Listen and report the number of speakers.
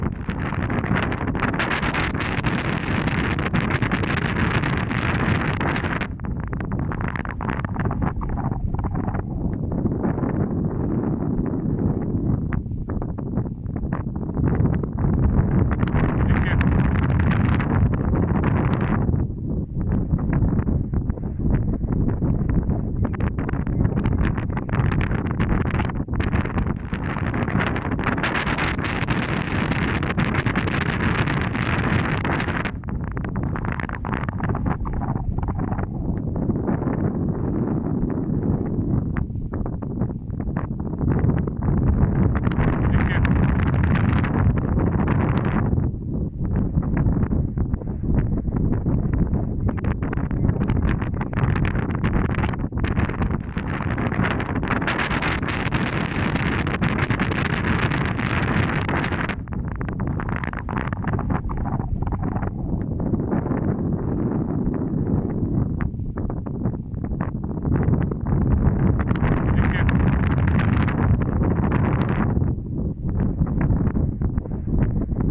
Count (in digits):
0